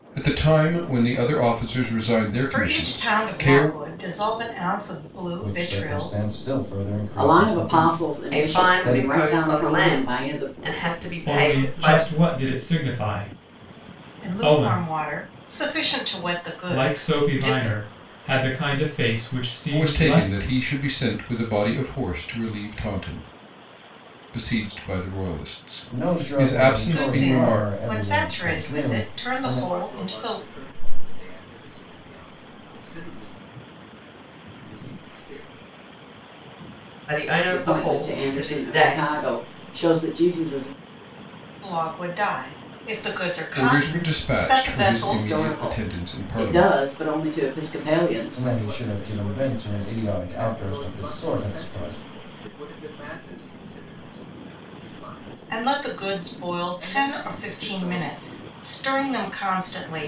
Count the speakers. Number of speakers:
seven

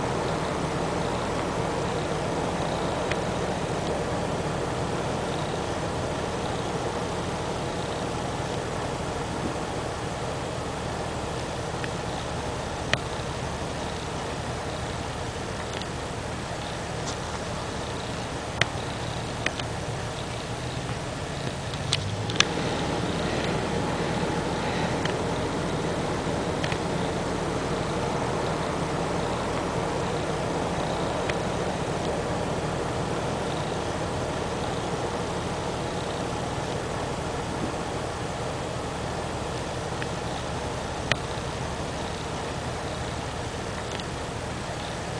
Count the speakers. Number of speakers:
zero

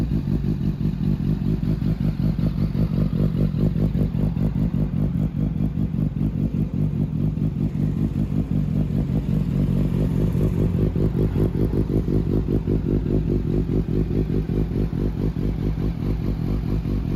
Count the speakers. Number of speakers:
zero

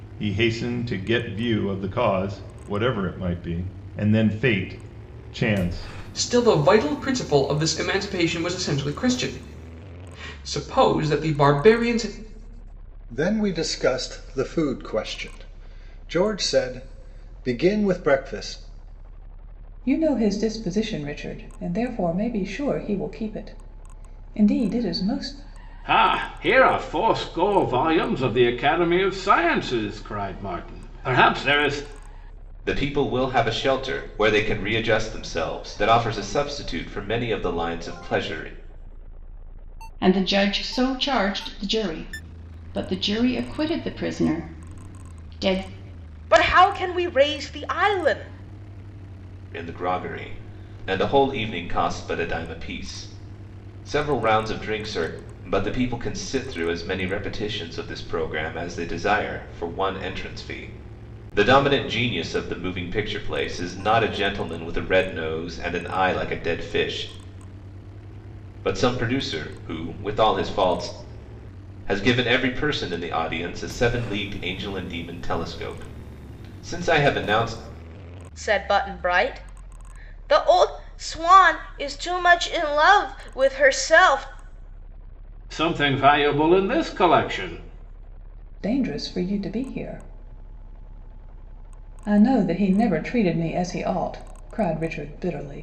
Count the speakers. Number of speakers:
eight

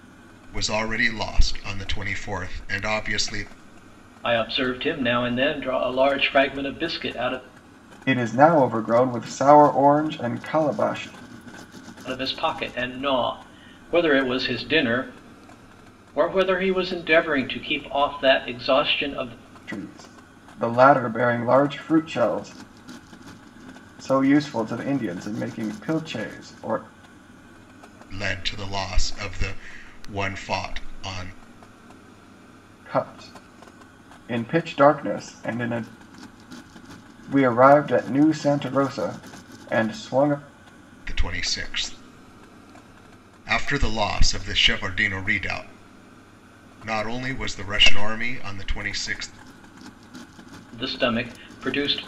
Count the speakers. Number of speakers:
three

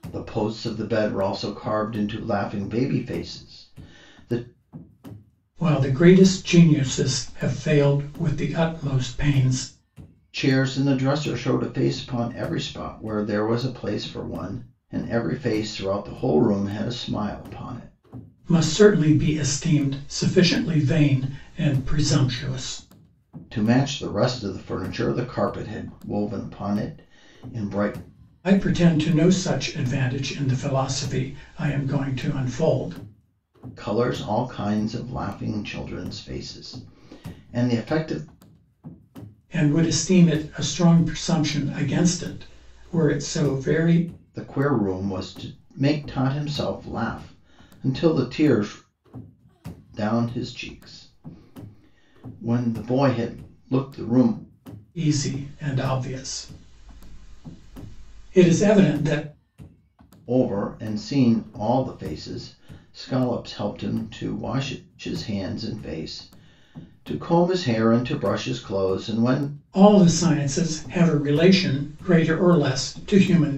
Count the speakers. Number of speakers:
two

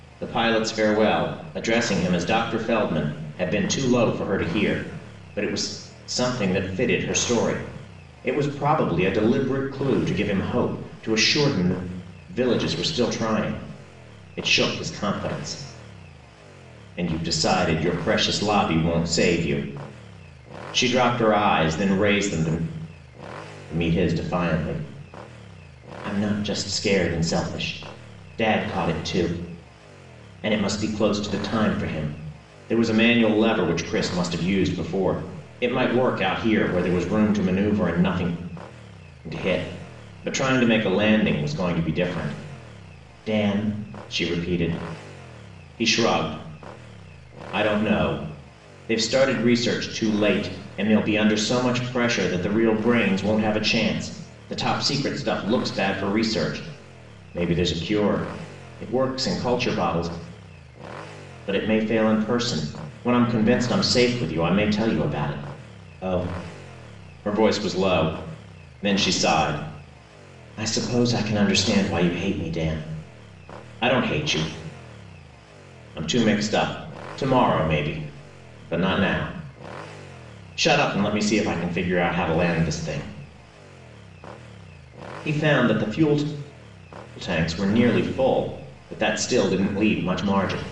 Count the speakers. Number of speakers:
one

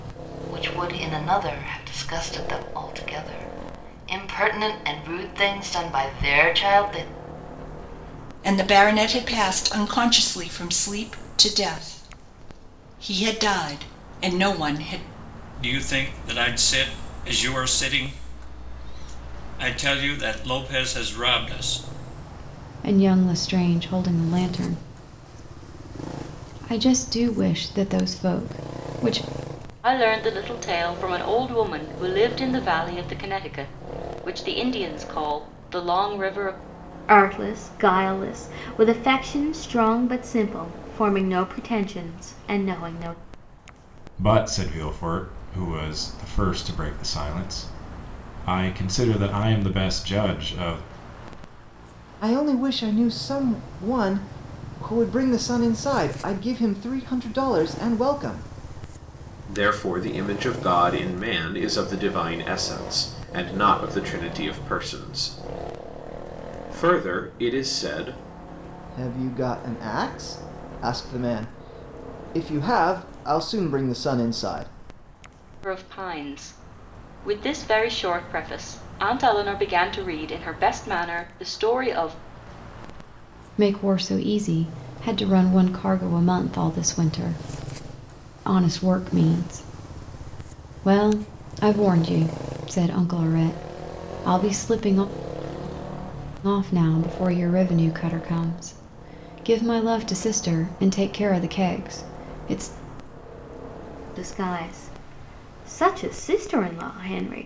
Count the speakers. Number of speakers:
nine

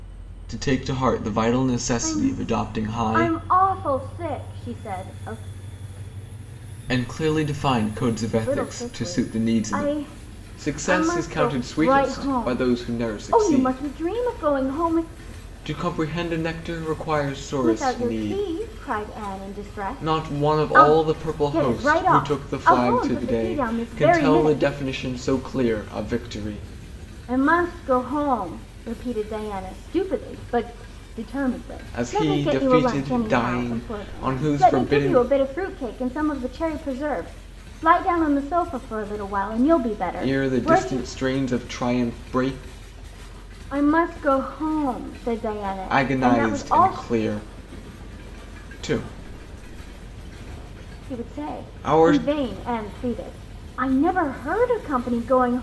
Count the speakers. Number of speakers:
two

